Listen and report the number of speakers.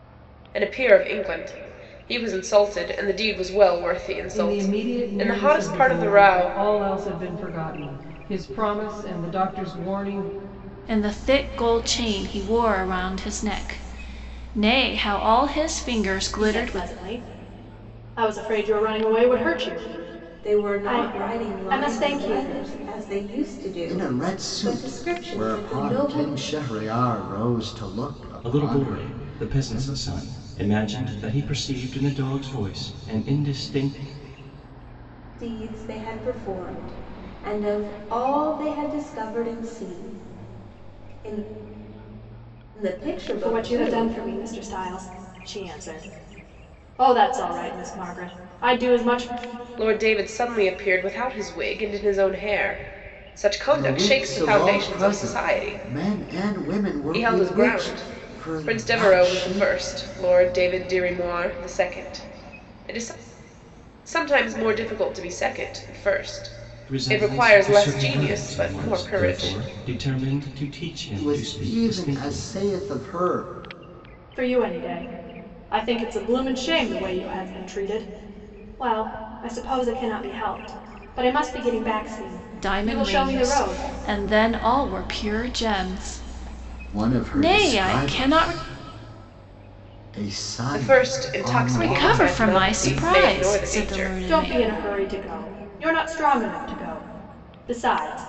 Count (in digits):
7